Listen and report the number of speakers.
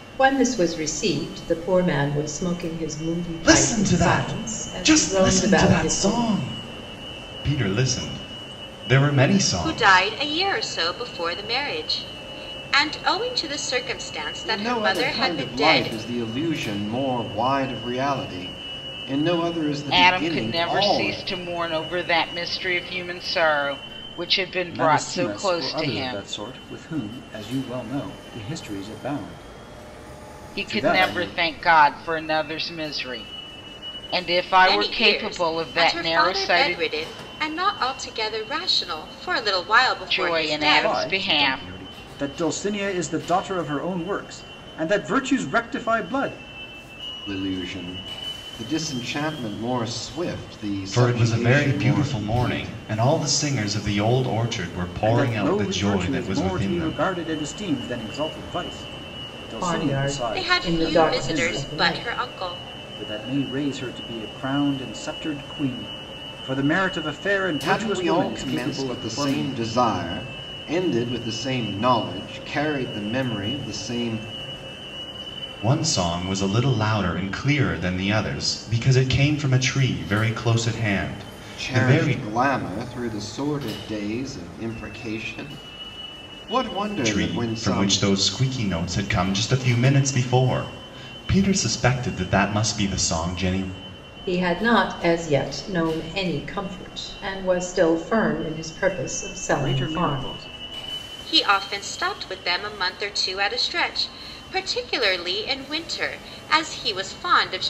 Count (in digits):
6